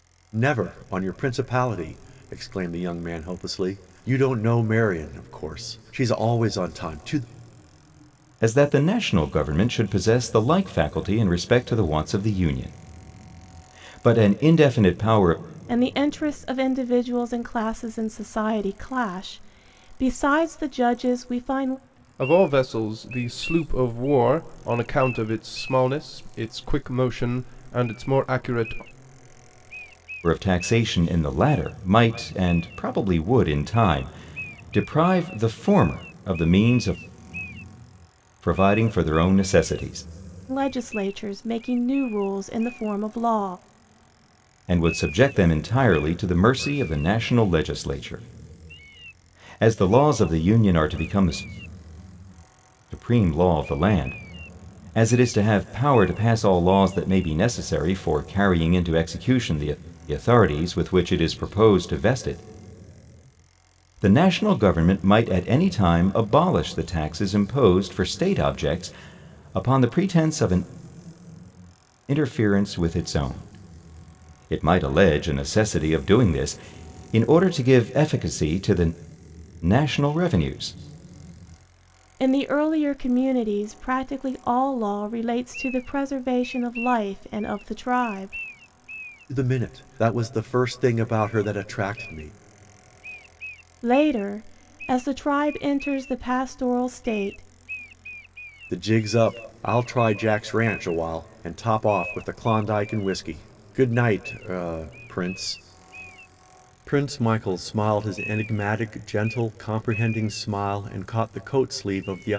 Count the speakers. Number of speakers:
4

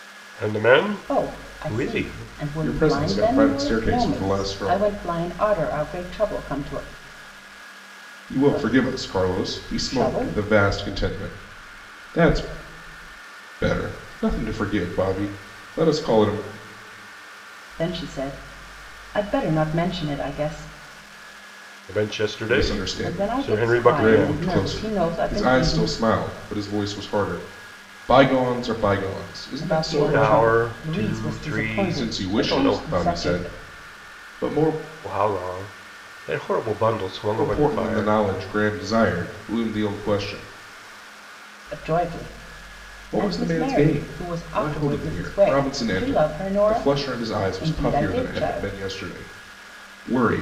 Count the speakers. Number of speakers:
3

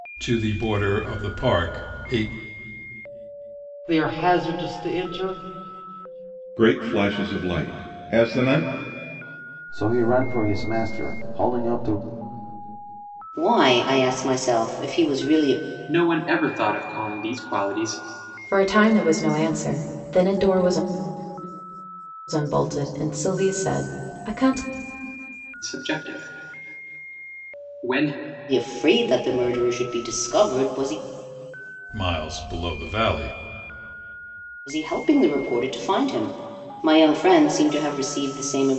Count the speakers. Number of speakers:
7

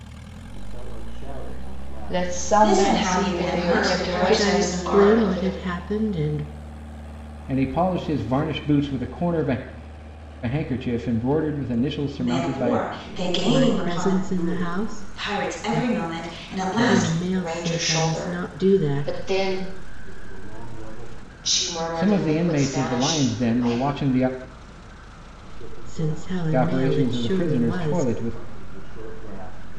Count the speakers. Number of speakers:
6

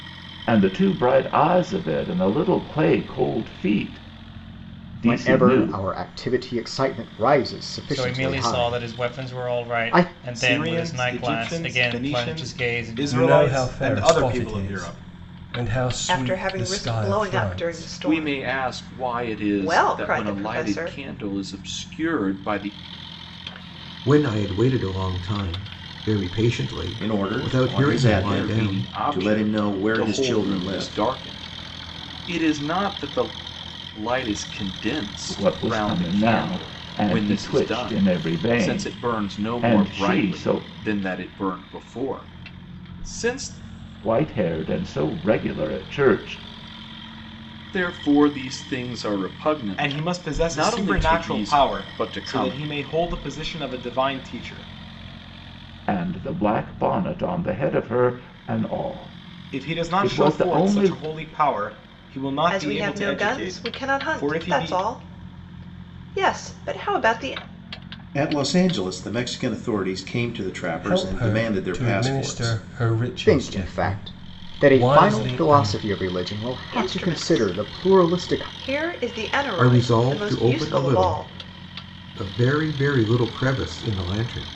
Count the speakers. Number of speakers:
9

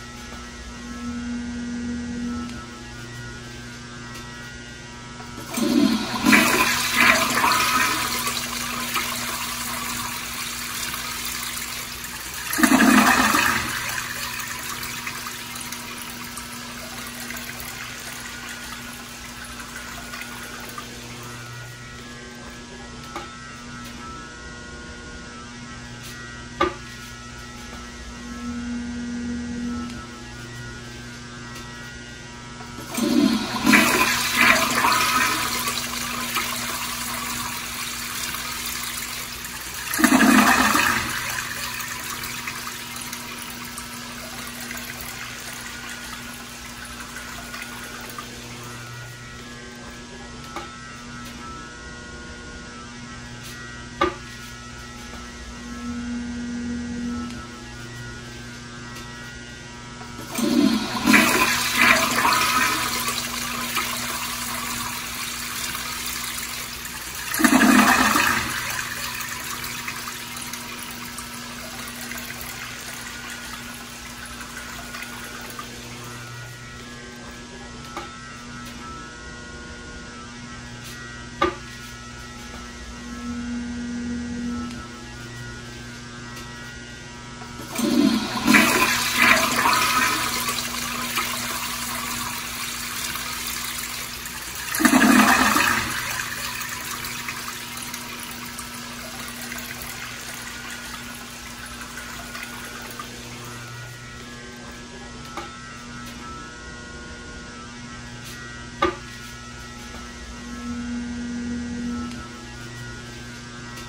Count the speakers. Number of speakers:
0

